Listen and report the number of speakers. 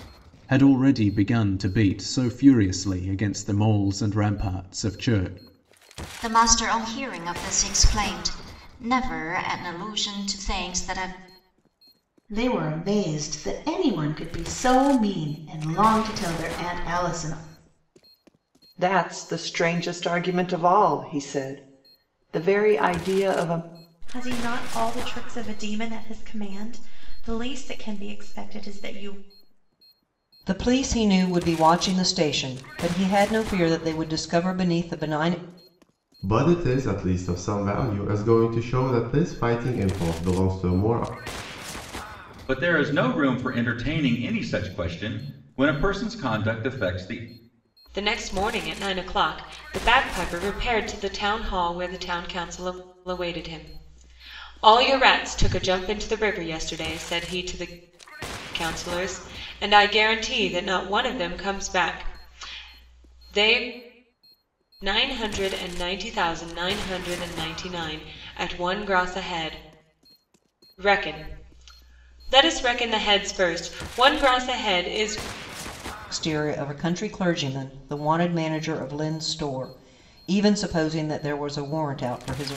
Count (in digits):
9